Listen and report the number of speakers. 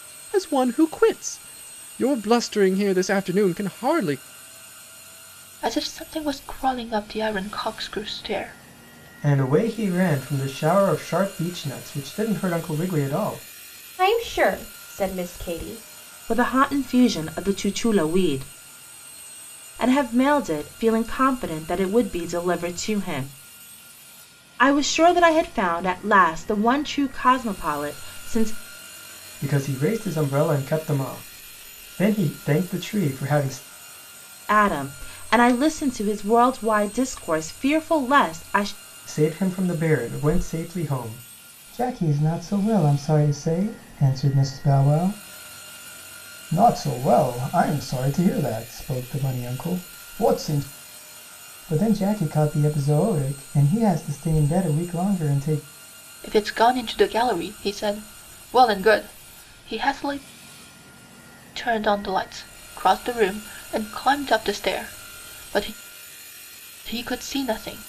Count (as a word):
five